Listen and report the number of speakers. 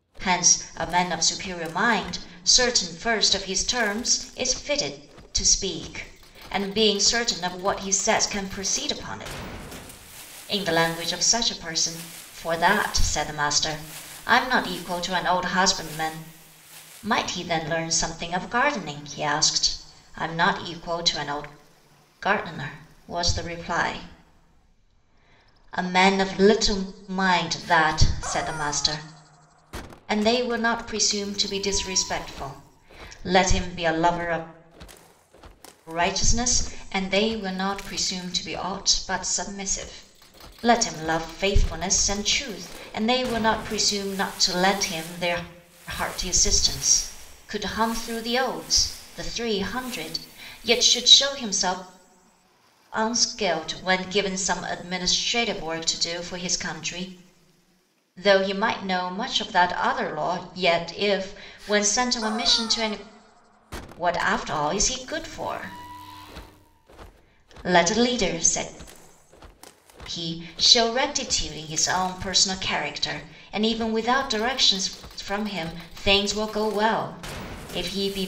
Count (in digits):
1